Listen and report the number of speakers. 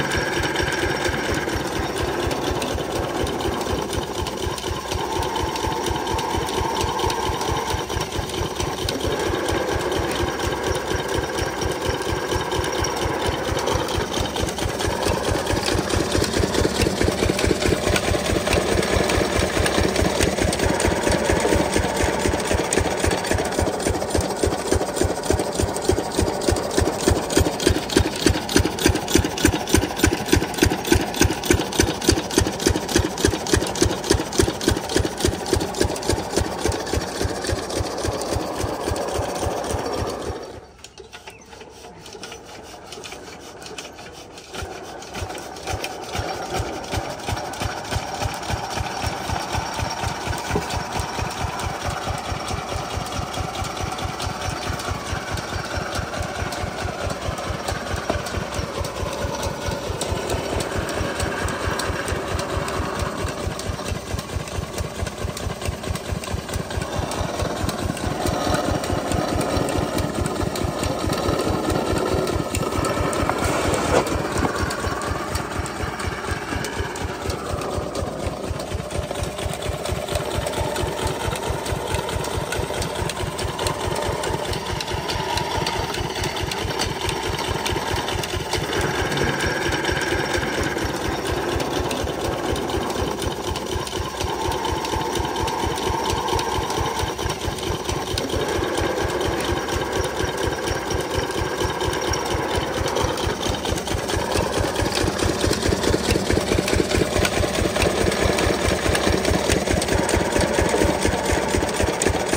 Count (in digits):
0